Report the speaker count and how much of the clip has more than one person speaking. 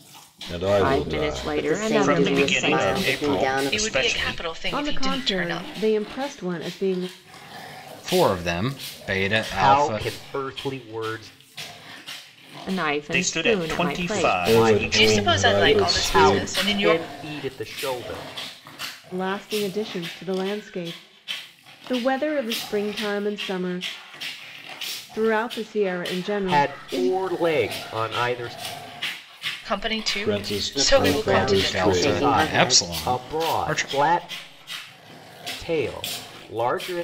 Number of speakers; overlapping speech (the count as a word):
eight, about 37%